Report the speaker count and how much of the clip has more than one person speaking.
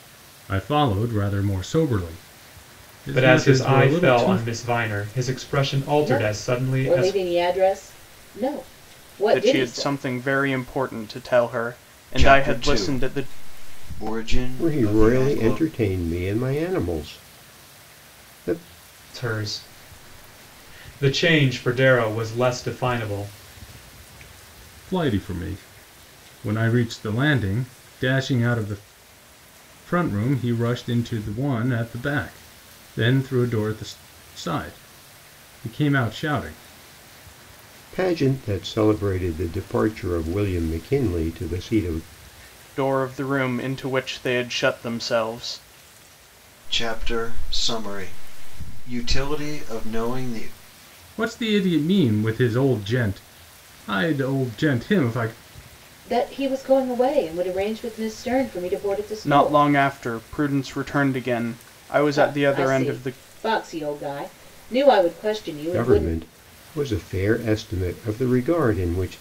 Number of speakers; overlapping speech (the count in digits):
6, about 11%